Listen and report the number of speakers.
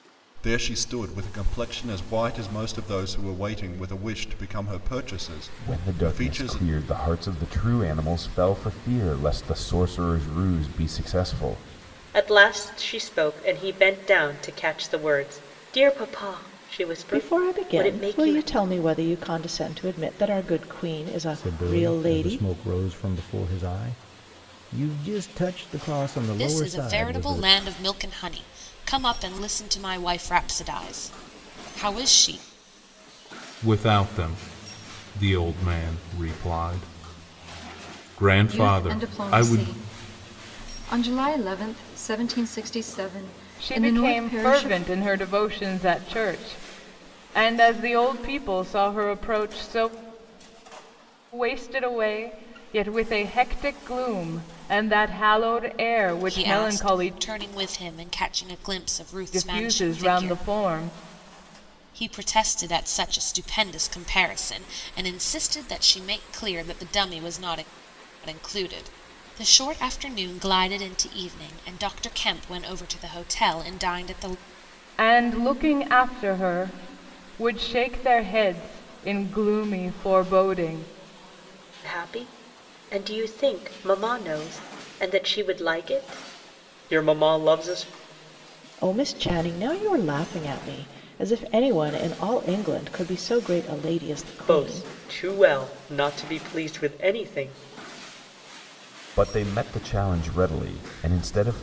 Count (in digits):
9